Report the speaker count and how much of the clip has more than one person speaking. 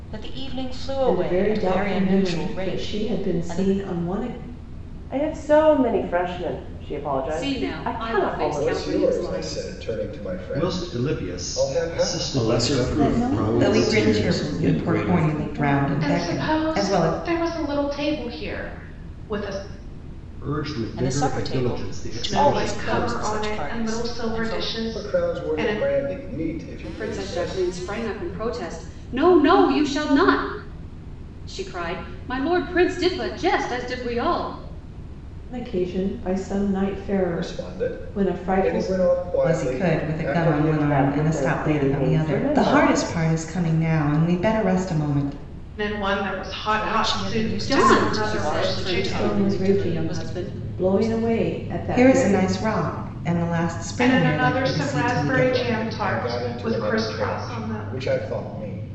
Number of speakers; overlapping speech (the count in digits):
10, about 54%